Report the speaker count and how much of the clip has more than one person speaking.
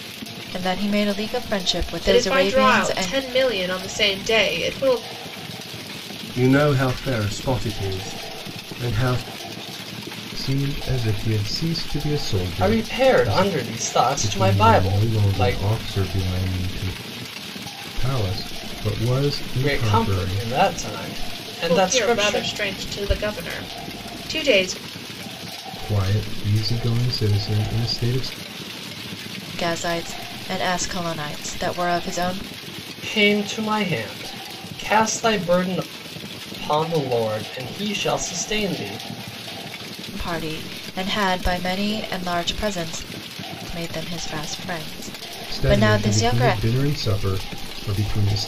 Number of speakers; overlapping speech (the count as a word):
five, about 14%